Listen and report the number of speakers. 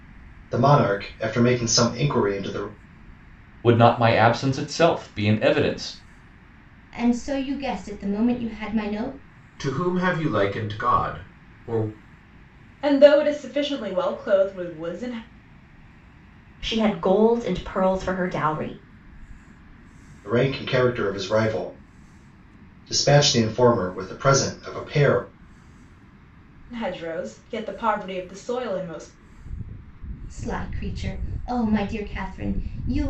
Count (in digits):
6